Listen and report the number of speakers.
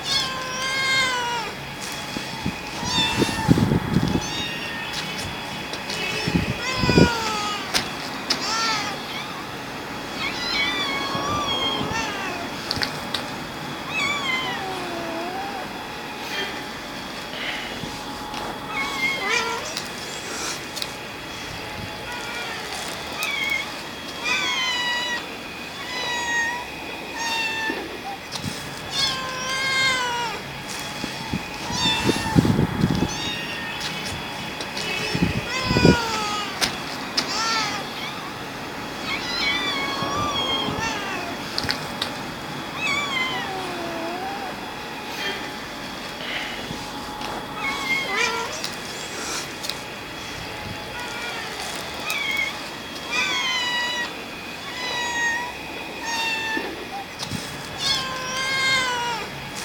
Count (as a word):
zero